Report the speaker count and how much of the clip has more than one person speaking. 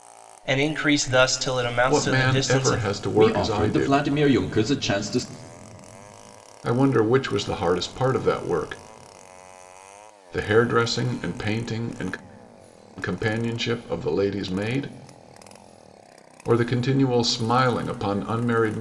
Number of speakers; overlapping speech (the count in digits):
3, about 10%